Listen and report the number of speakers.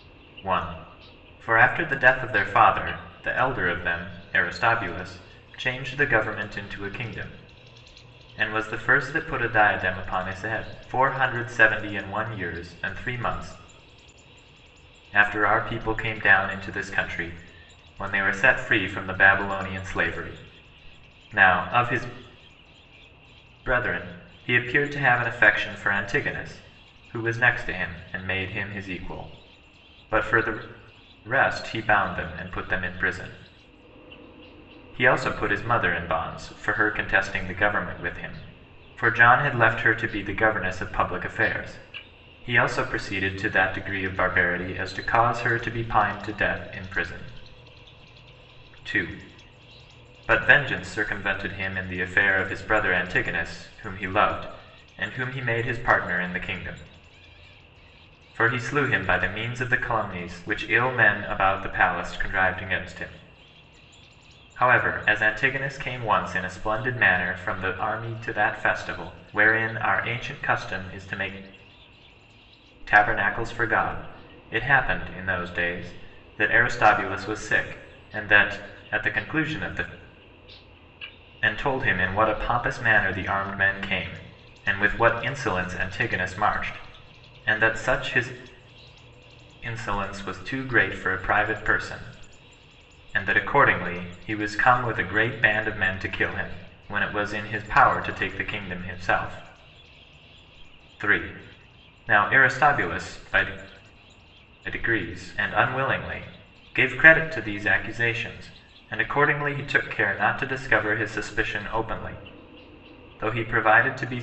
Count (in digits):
1